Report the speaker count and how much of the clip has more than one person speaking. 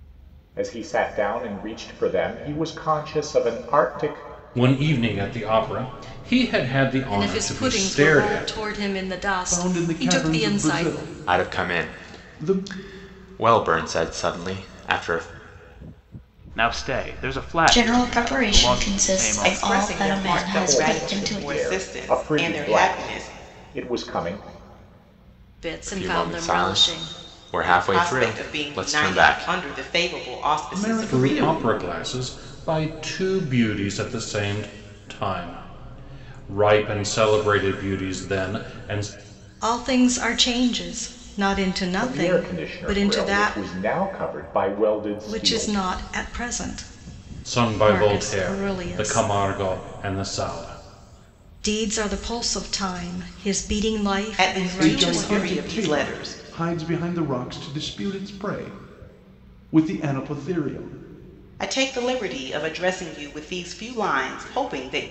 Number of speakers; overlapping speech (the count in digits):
8, about 31%